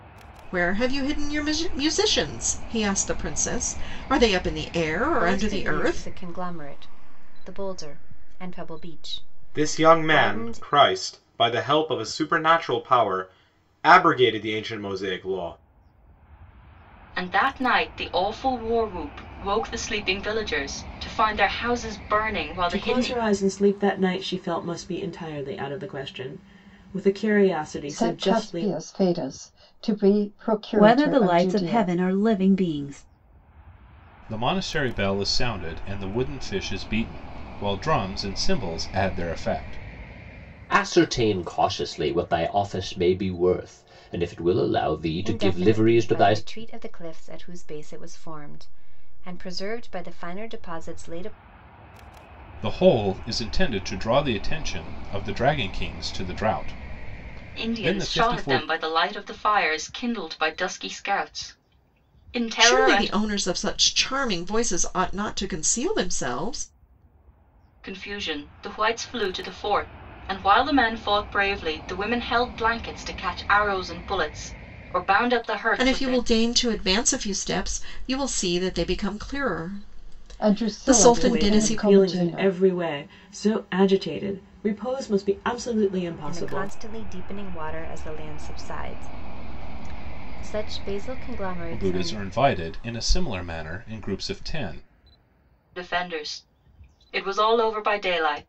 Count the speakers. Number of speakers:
9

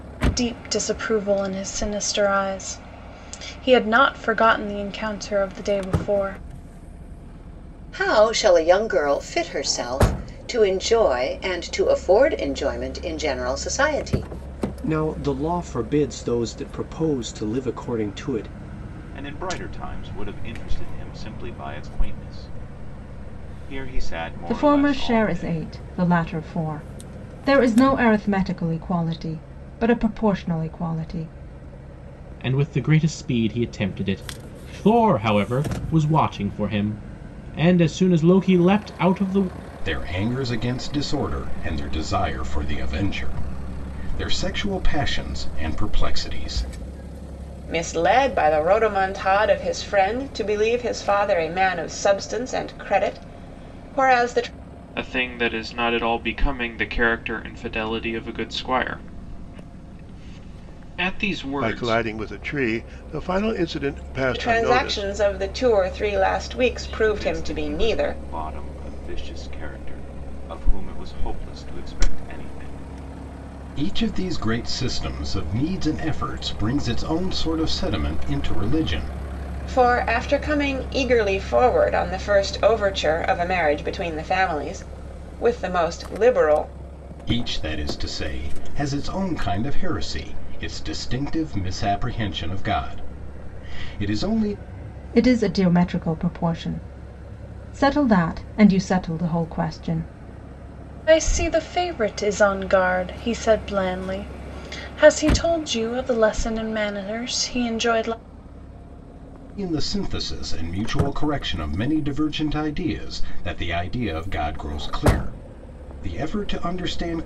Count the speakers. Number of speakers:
10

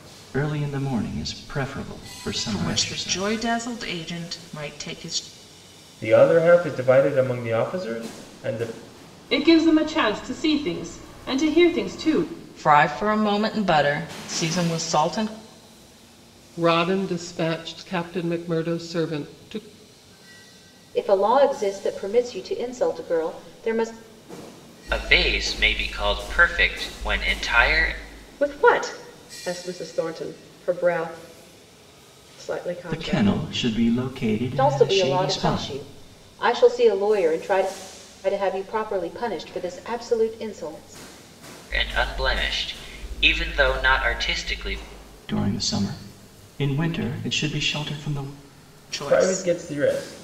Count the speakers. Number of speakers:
9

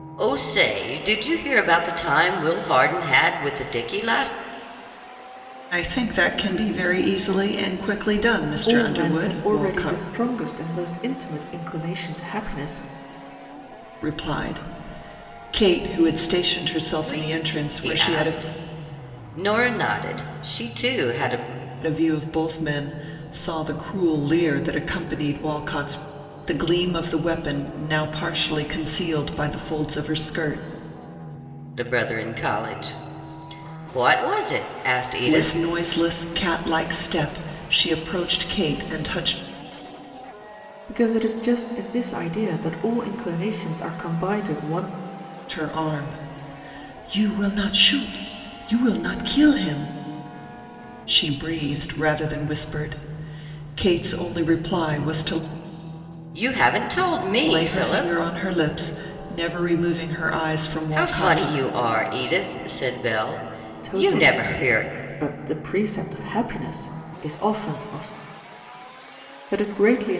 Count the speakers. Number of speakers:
3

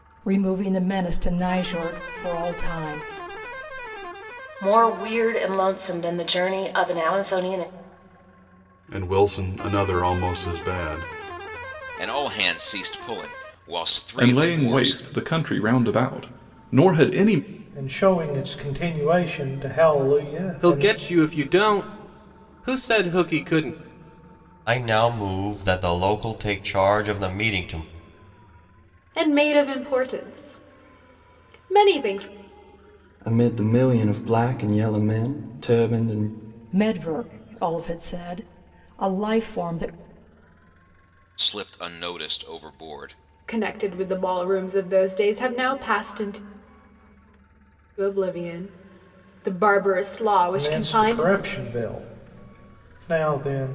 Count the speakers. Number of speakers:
10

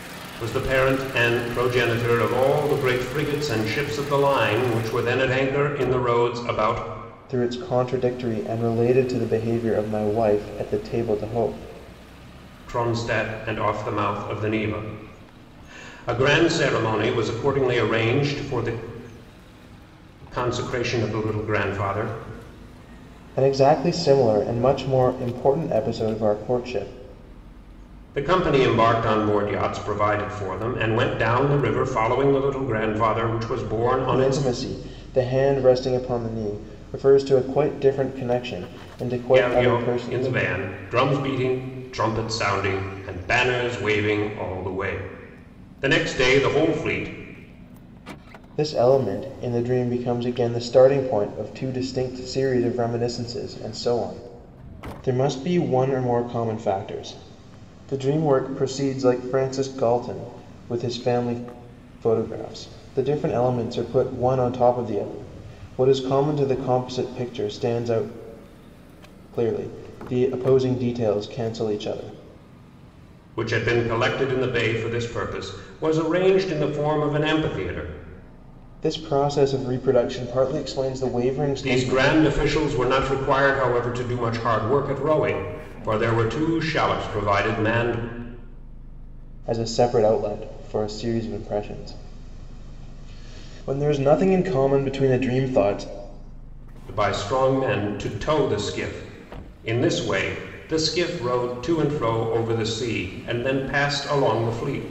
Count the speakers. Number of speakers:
2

